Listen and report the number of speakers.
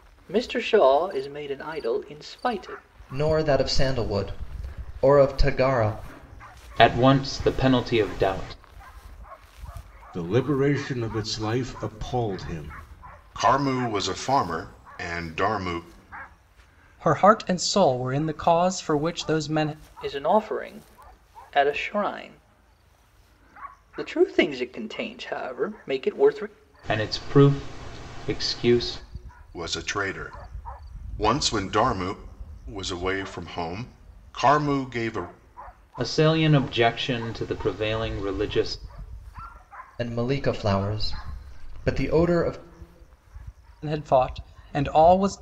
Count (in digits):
6